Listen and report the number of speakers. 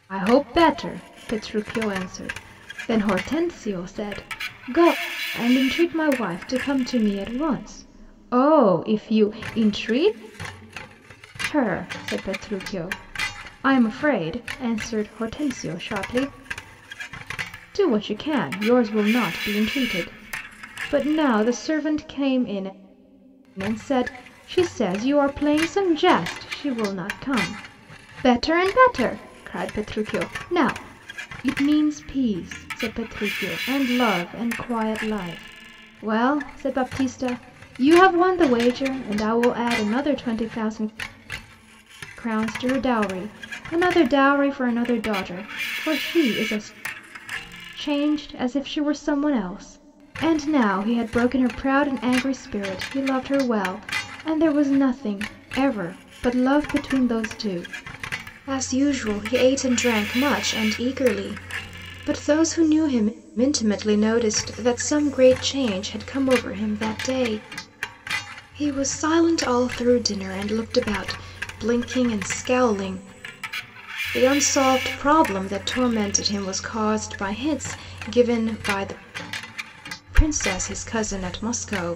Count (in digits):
1